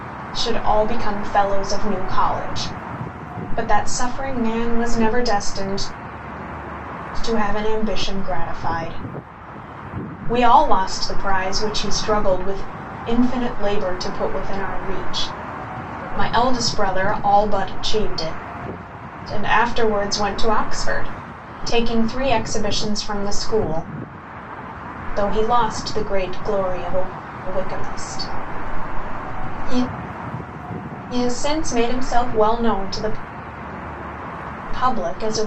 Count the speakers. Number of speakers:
one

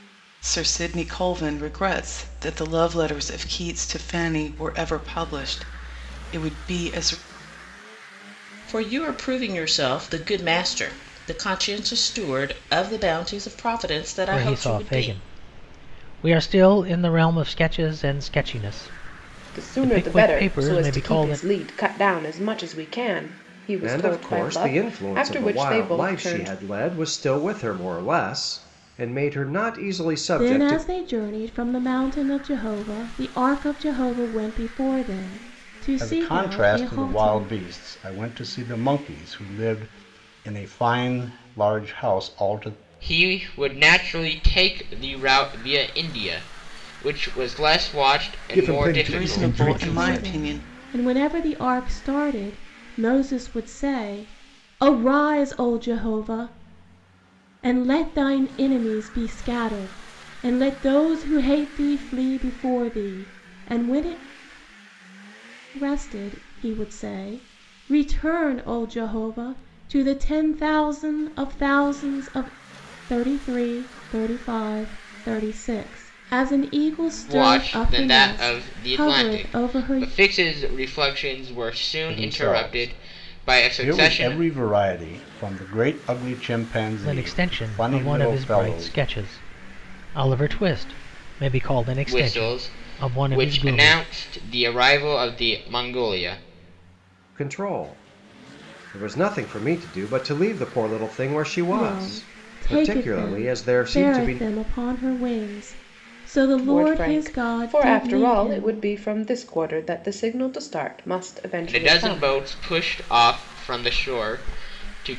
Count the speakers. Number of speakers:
nine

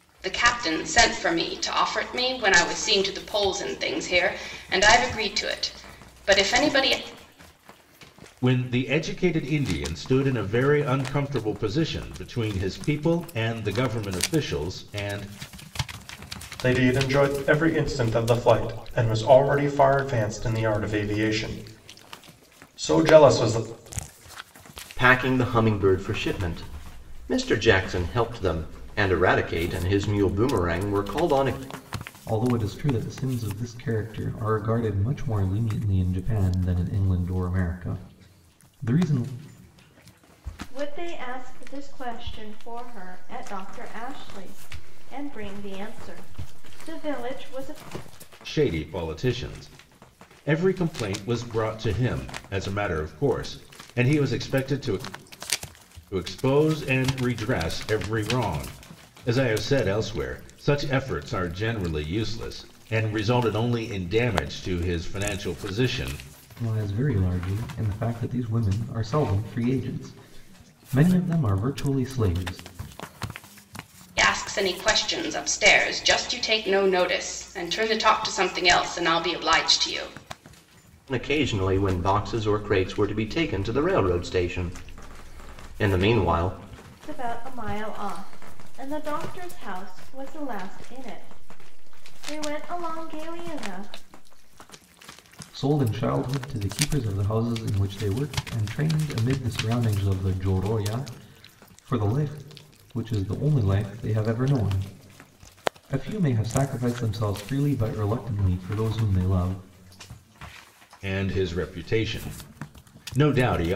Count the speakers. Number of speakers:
six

